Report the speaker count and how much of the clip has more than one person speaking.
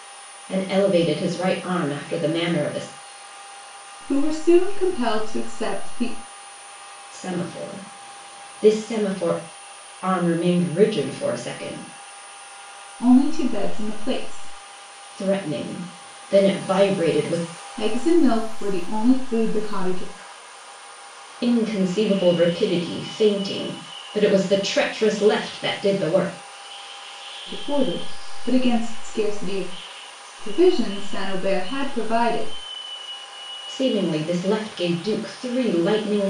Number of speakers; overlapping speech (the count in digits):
2, no overlap